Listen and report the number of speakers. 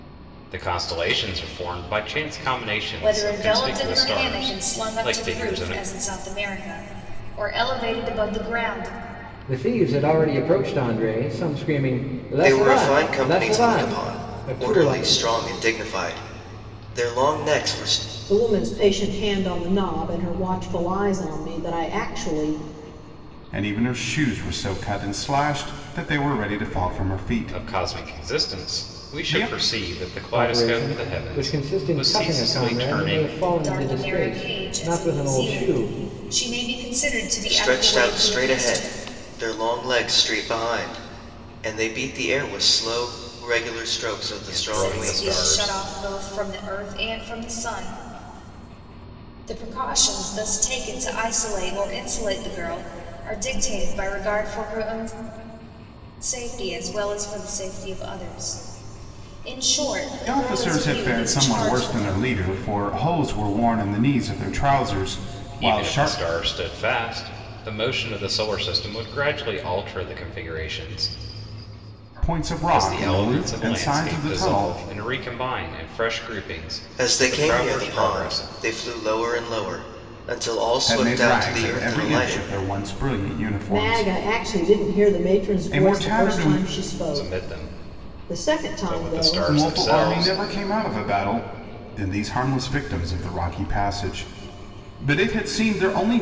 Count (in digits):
6